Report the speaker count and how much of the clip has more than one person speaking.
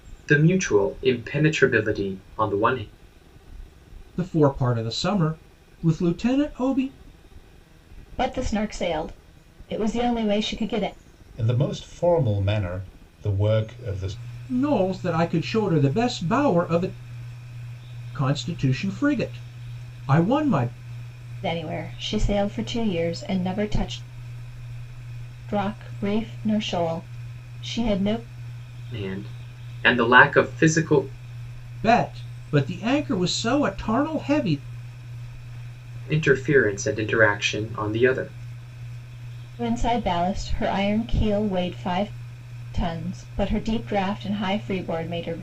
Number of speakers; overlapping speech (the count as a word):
four, no overlap